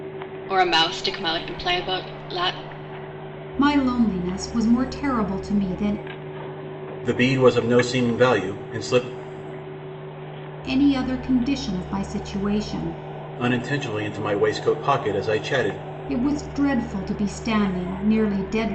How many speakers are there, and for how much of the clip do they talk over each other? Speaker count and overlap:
3, no overlap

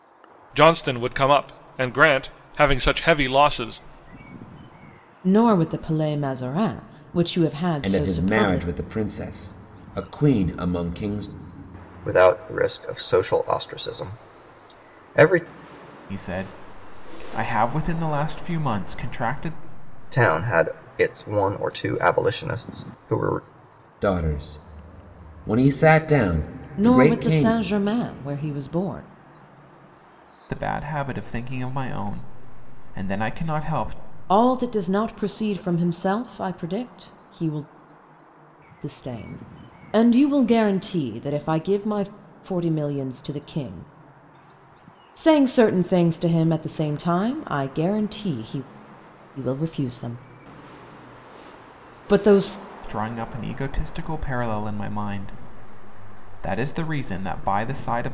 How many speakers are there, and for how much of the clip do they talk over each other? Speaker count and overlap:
5, about 3%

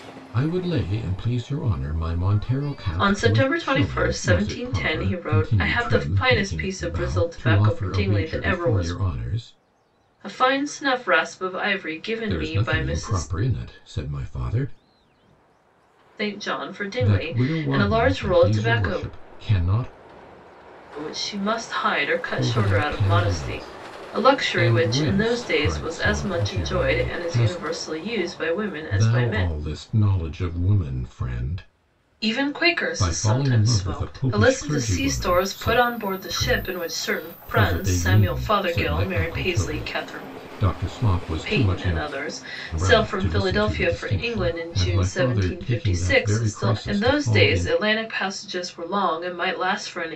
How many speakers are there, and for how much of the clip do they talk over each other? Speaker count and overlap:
2, about 54%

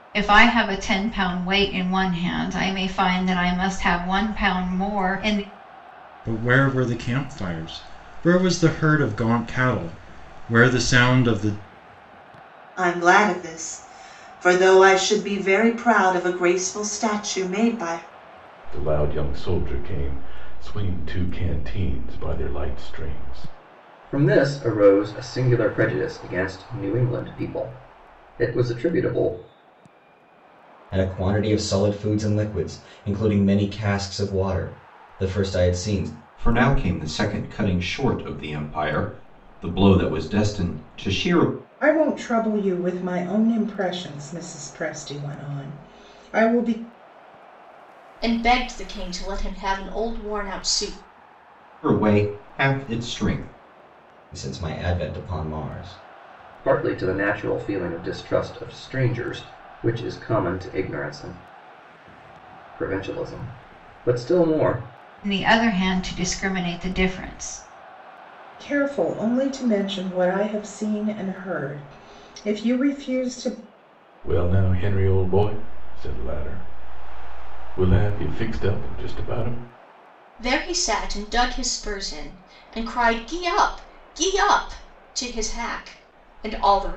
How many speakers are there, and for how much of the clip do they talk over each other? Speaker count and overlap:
9, no overlap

